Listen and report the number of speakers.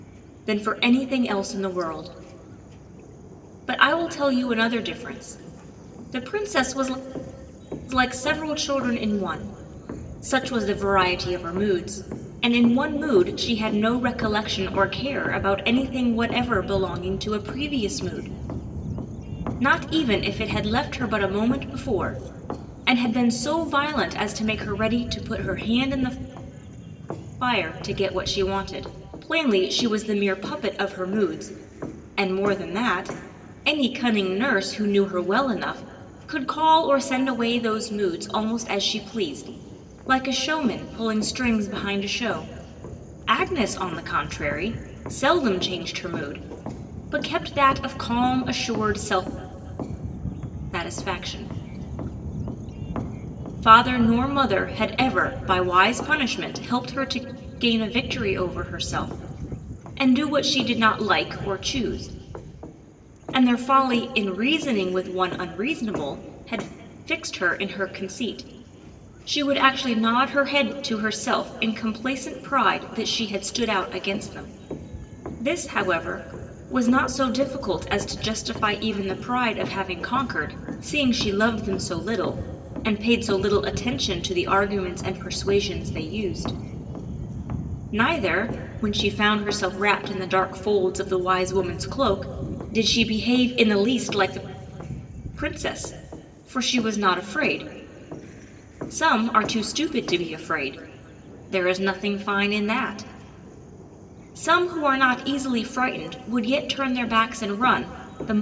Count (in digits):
1